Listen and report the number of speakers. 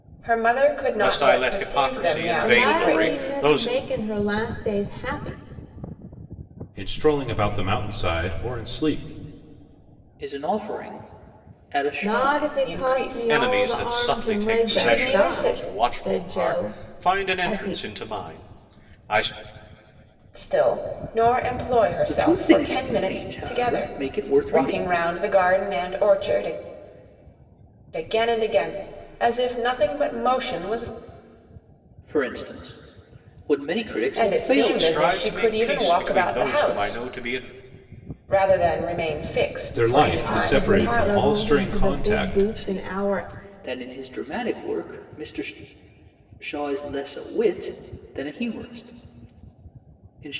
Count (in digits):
5